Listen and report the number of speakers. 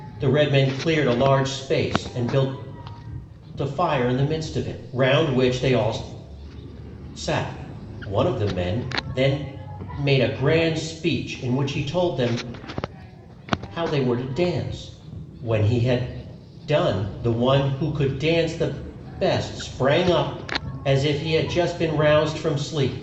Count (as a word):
one